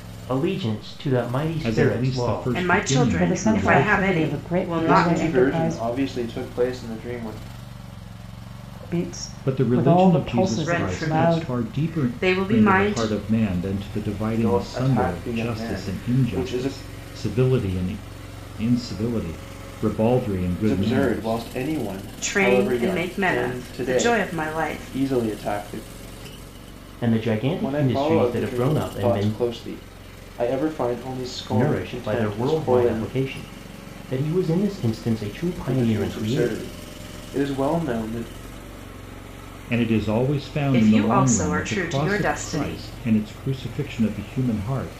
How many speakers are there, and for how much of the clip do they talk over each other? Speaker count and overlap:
5, about 45%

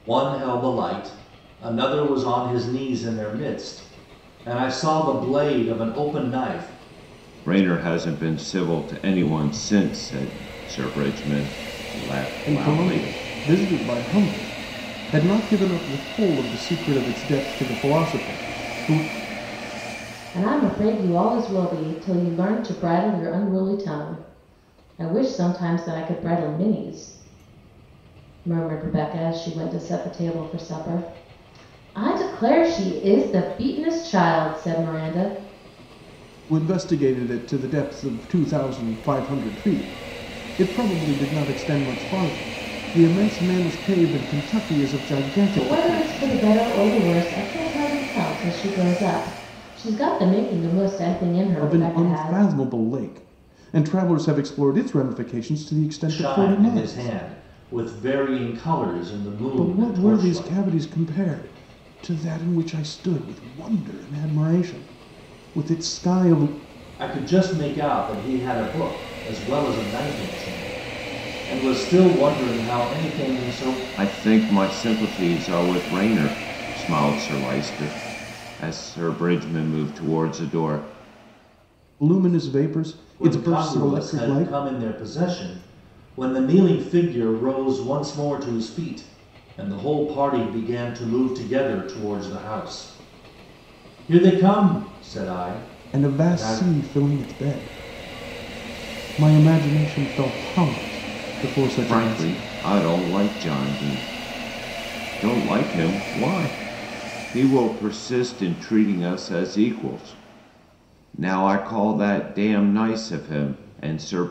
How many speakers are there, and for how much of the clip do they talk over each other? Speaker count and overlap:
4, about 7%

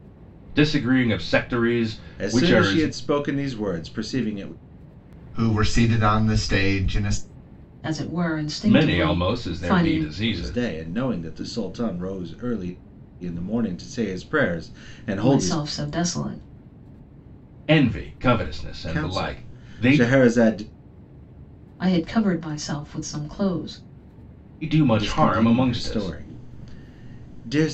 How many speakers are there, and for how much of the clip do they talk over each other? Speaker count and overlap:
4, about 20%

